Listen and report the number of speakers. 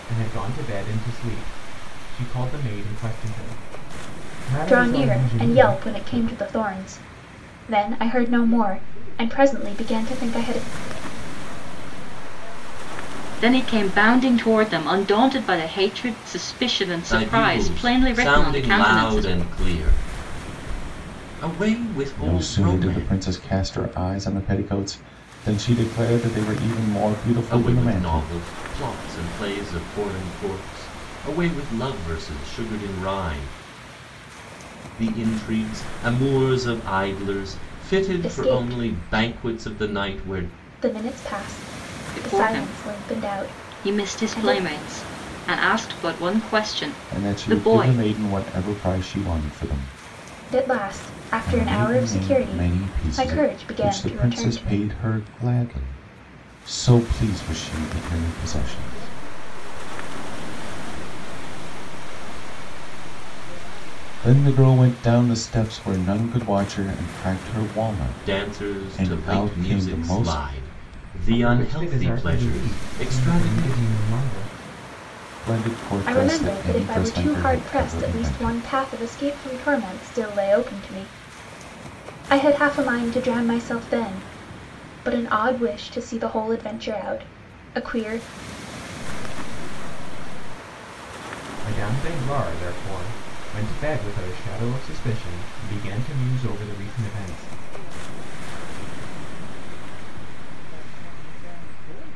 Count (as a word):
six